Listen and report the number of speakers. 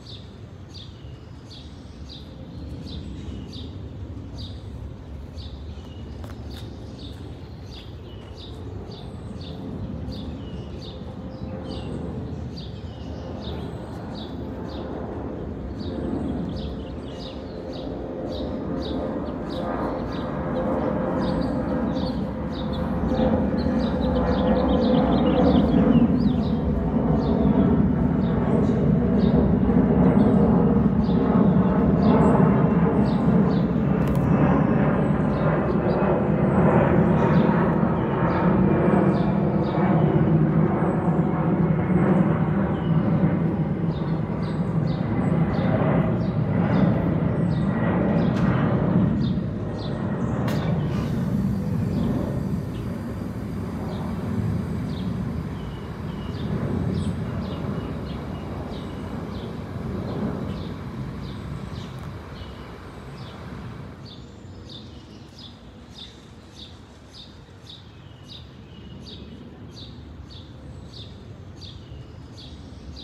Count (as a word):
zero